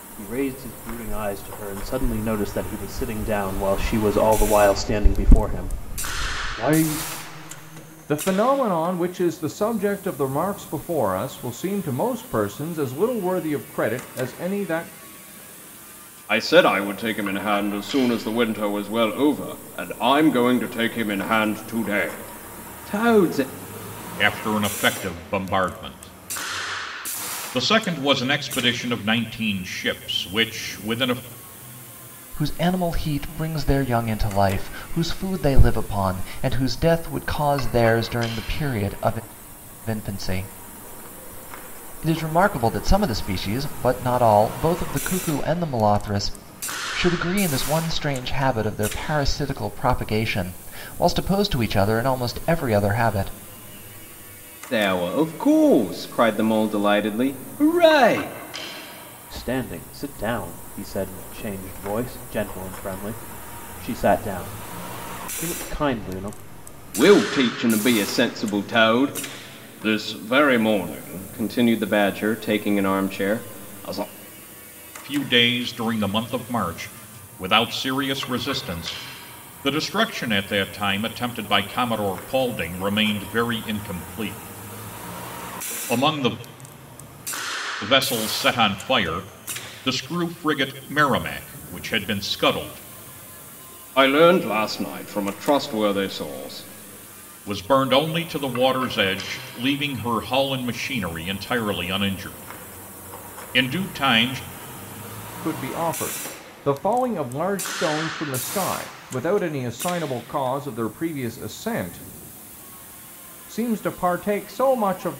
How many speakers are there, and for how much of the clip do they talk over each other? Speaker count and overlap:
5, no overlap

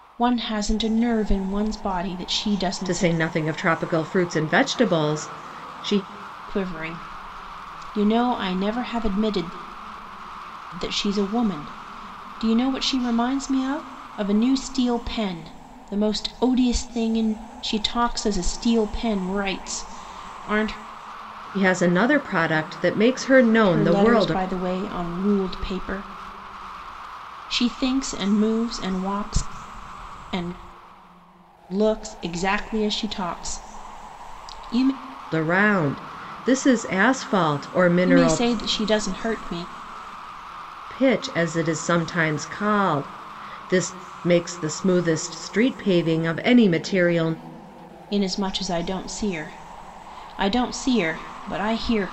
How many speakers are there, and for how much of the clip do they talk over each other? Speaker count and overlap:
2, about 3%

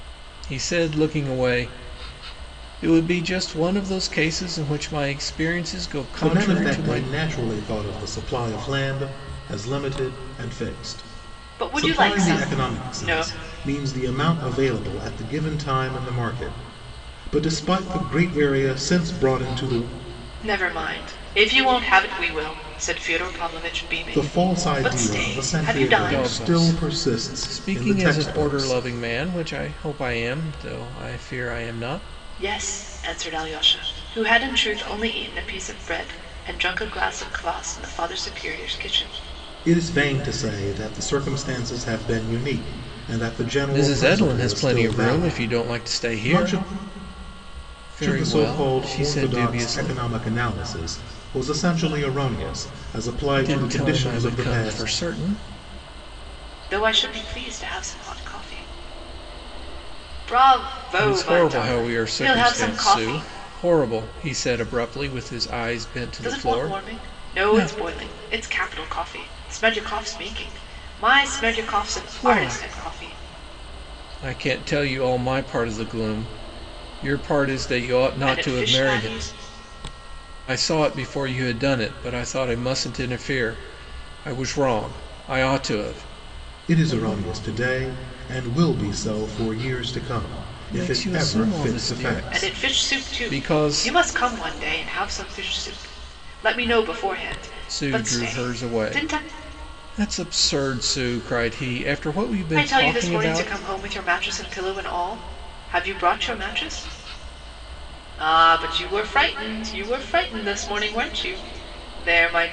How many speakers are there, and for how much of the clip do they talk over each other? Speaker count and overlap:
3, about 23%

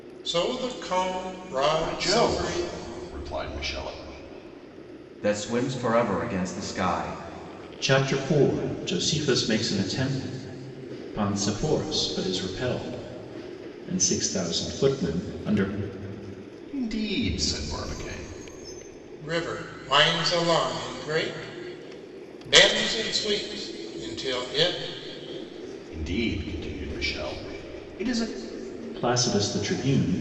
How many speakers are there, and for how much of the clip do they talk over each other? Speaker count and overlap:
4, about 3%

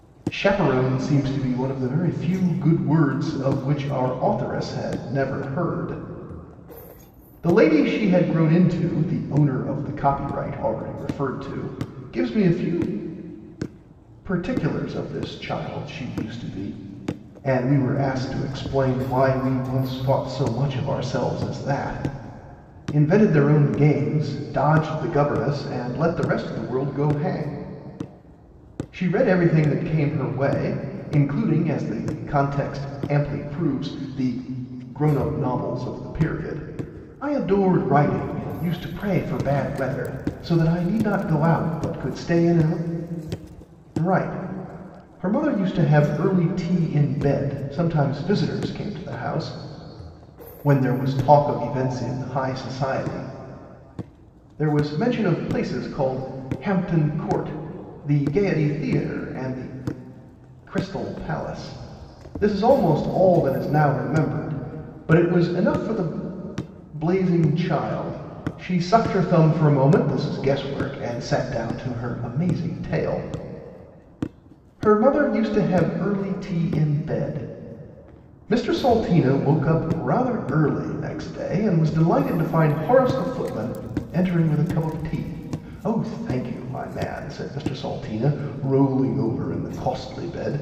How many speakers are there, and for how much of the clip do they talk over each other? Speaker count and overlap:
1, no overlap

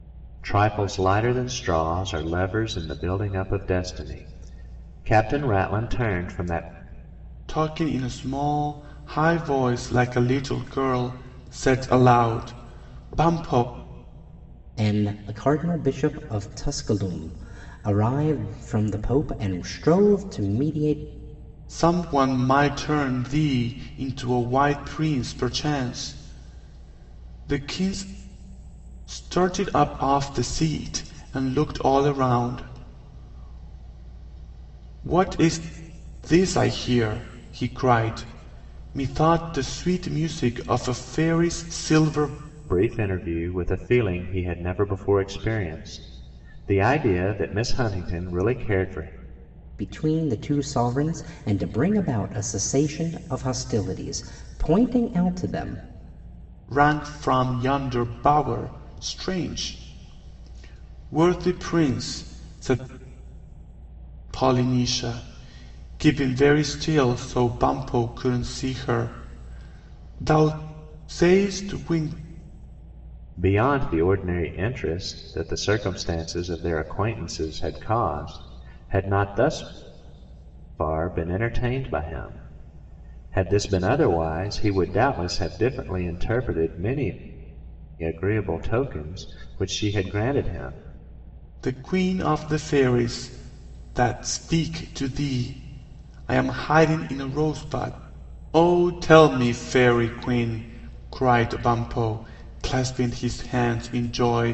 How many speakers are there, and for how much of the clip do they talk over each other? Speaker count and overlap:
3, no overlap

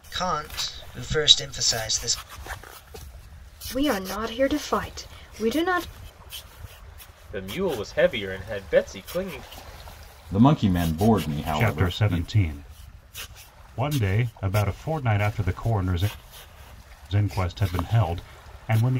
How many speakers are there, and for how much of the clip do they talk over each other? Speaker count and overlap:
5, about 4%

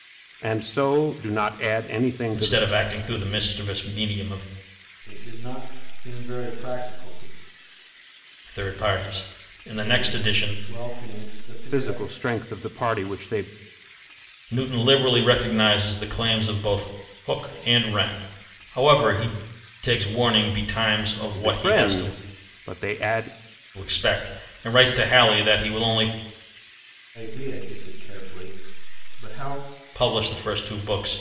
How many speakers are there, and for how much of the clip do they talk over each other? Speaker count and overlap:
3, about 8%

